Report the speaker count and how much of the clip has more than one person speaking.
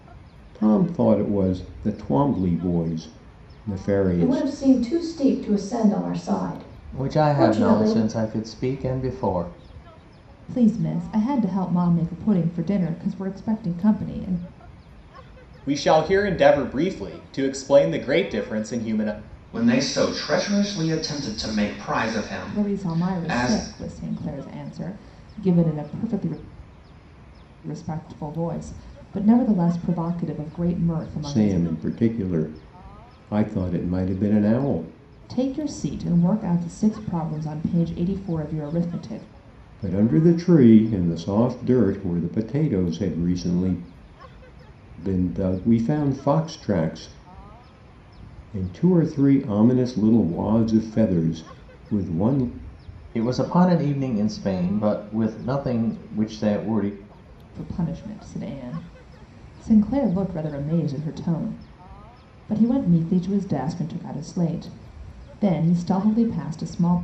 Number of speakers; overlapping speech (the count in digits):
6, about 4%